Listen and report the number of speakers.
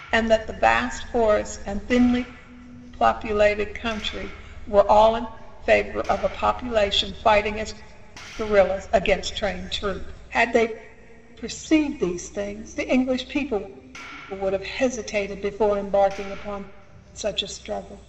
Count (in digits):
1